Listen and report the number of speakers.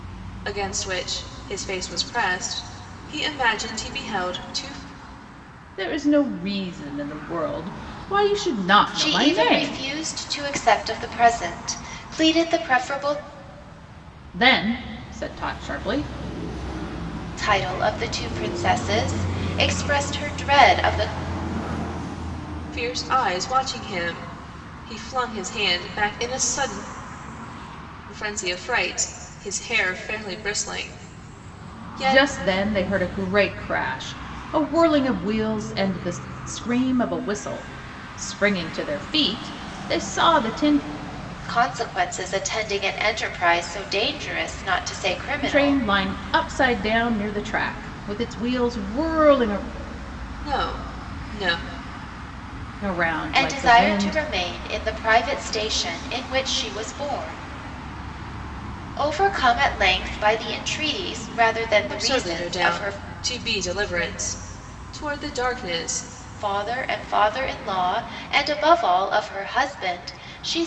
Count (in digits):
3